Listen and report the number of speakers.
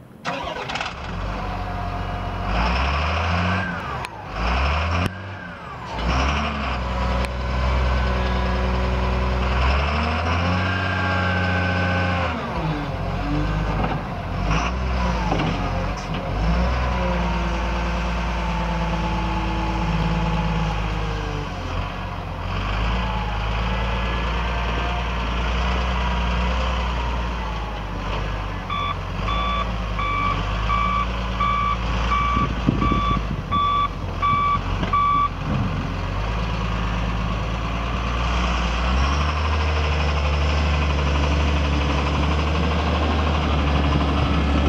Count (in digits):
0